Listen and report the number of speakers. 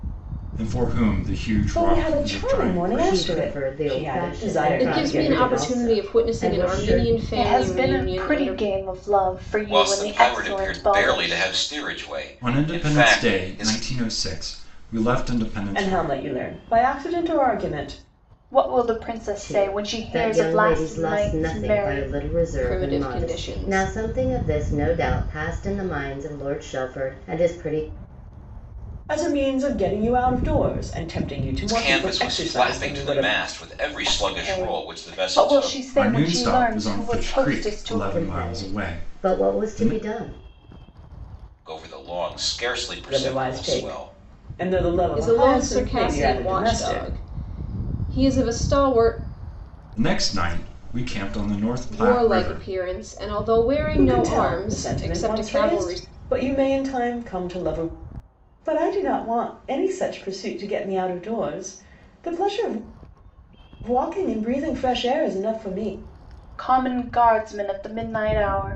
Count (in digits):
6